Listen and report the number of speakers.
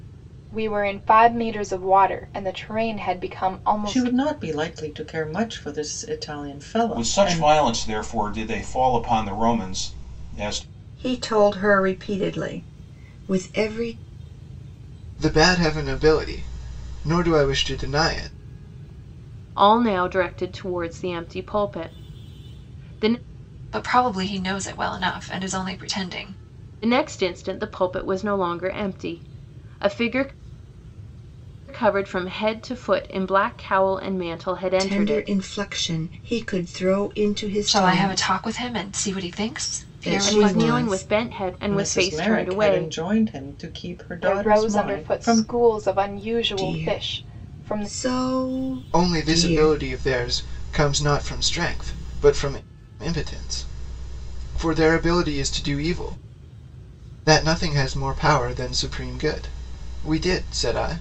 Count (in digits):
7